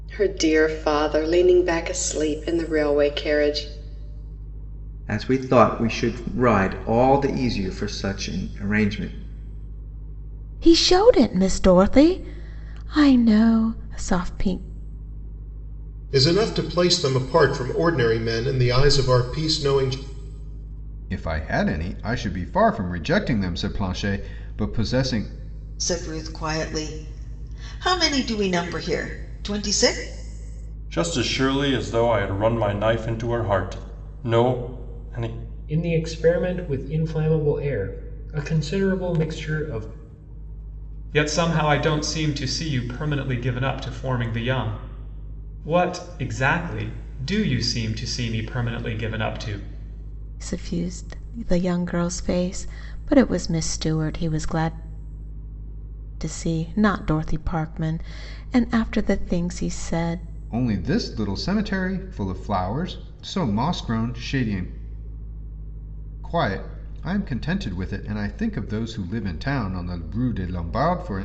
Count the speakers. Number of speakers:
9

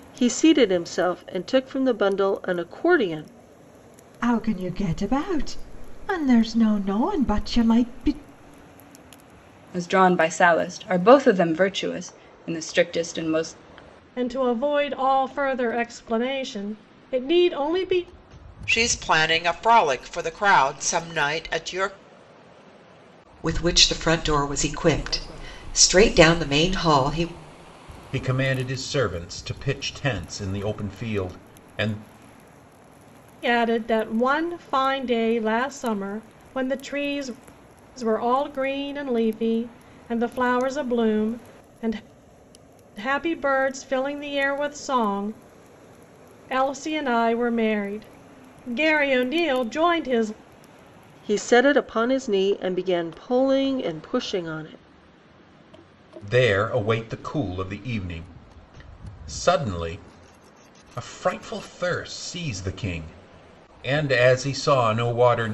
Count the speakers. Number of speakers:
7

